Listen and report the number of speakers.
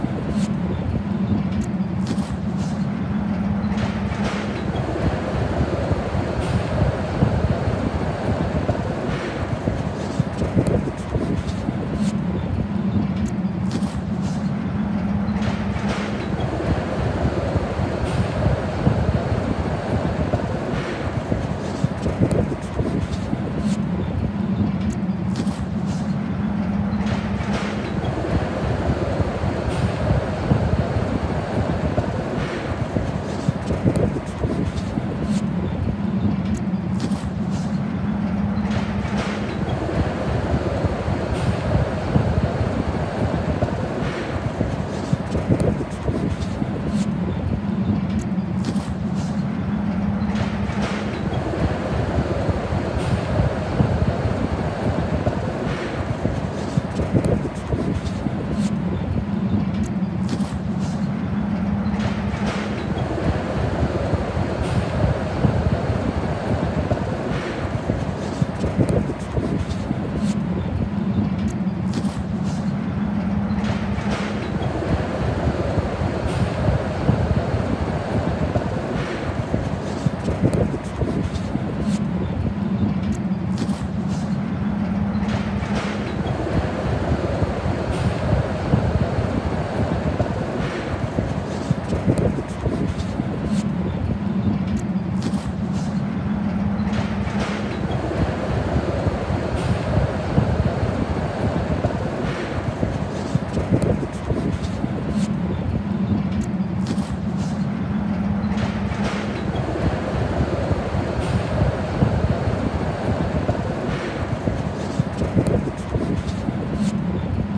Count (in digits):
0